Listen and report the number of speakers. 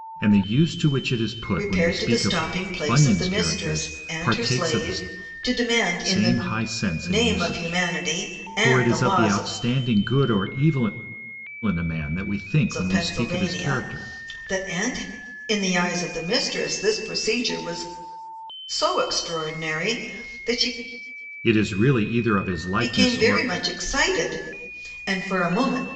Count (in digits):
2